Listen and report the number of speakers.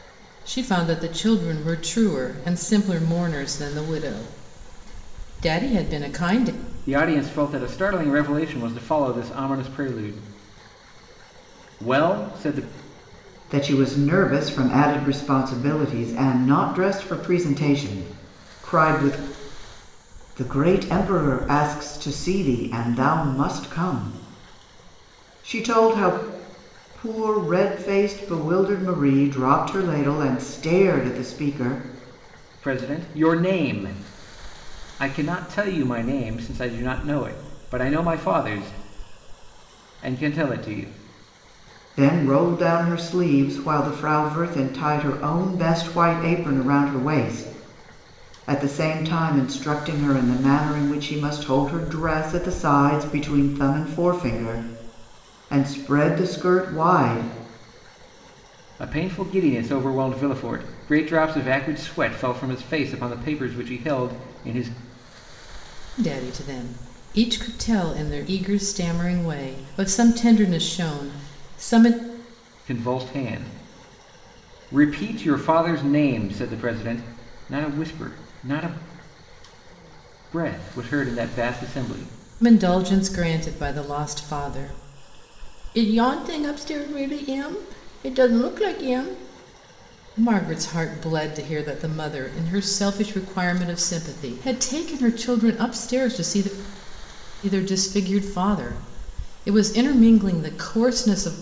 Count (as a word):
three